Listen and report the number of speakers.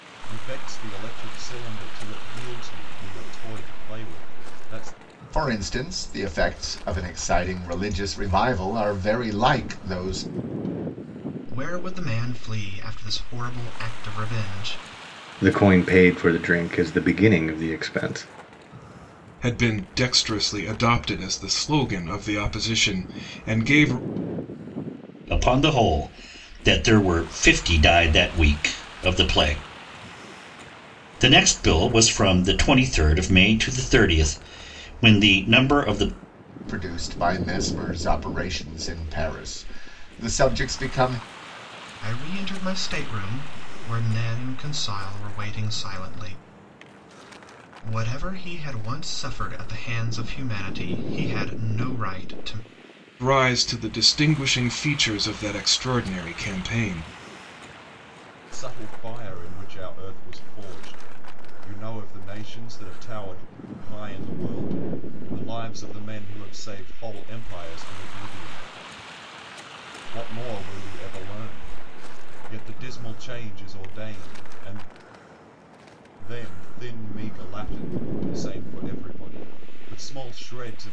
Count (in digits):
6